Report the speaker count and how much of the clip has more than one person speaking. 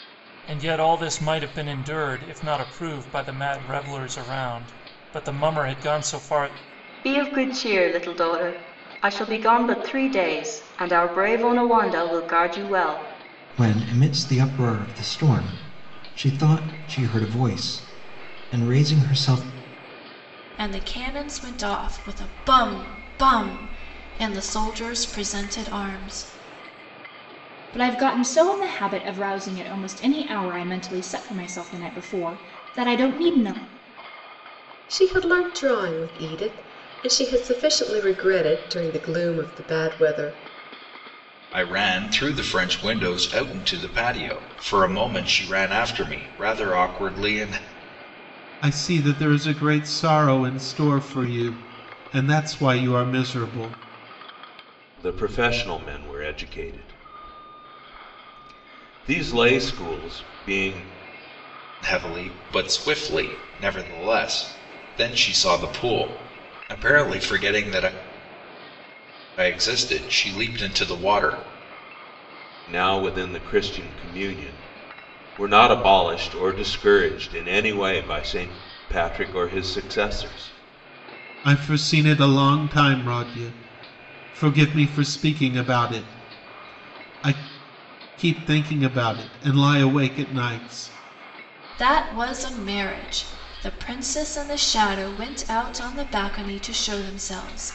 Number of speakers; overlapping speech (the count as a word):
nine, no overlap